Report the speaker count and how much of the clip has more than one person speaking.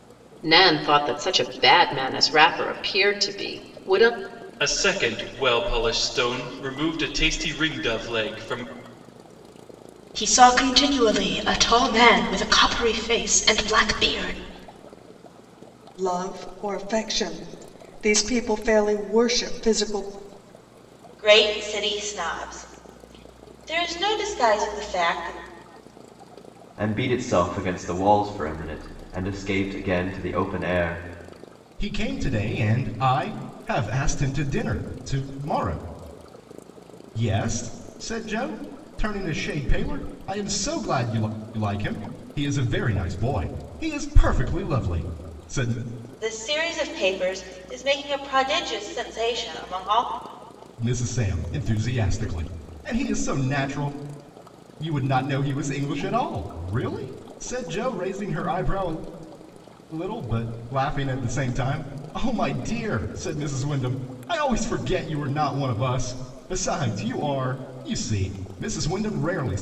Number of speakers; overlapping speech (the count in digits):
7, no overlap